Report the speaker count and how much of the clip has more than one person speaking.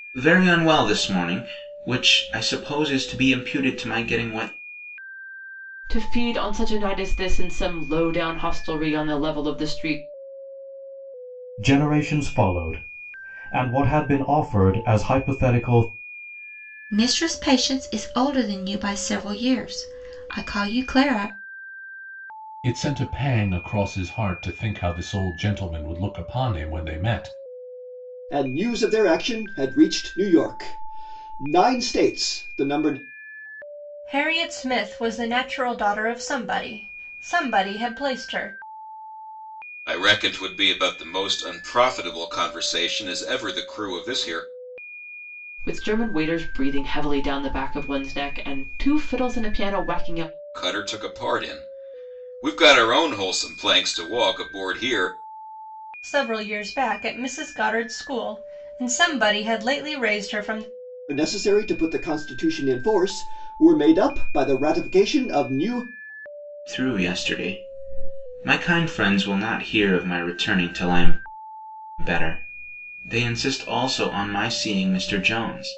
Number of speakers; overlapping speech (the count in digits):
8, no overlap